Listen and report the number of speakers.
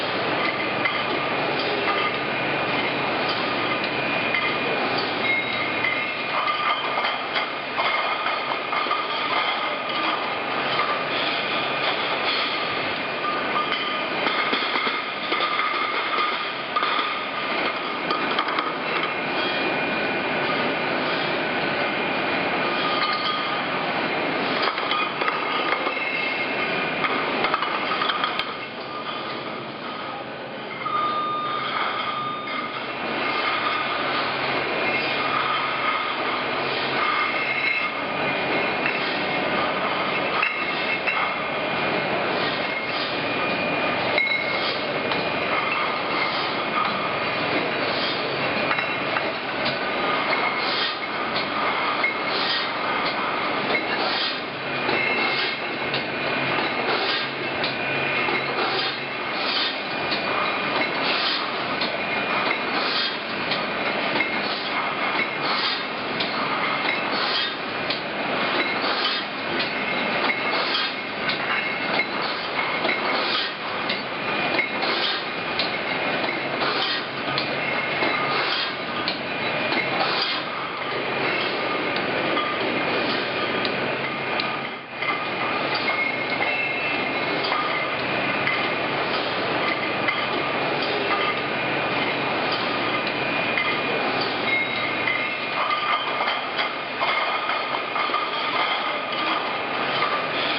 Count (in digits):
0